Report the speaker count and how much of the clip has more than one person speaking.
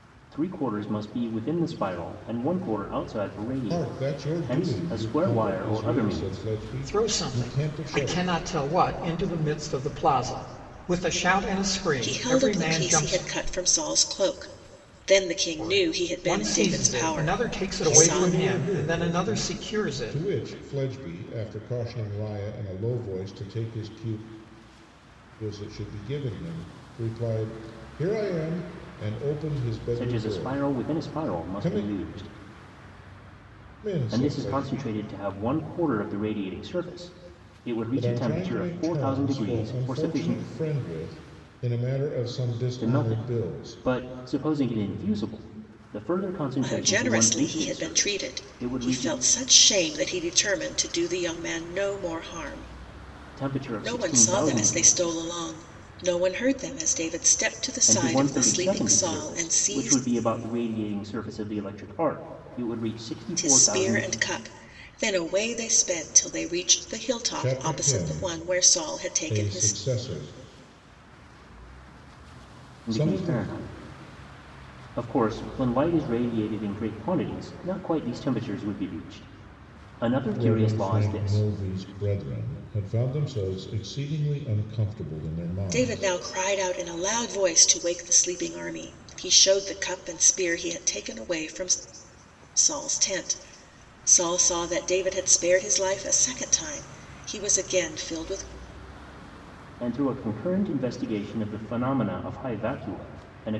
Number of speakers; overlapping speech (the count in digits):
4, about 27%